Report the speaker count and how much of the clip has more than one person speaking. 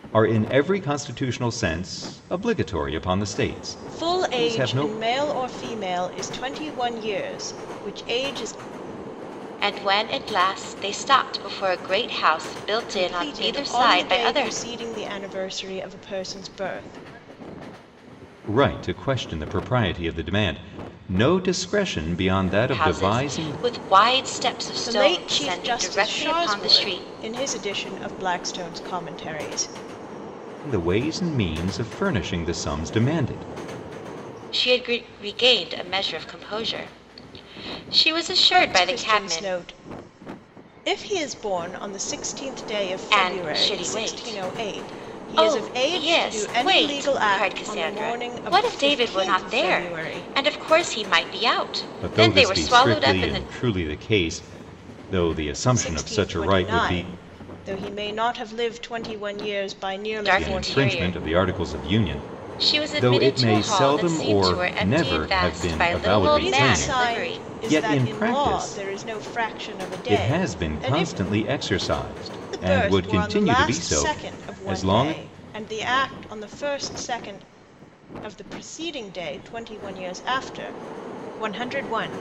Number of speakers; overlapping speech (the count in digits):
3, about 34%